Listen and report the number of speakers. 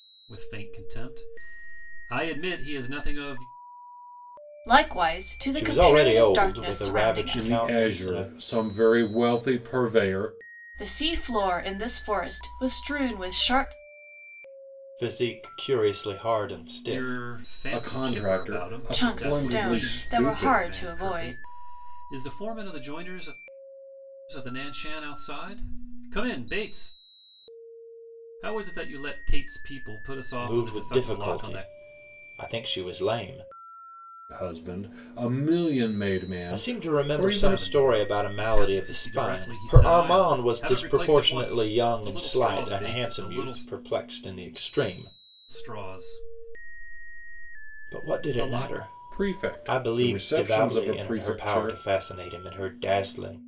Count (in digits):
4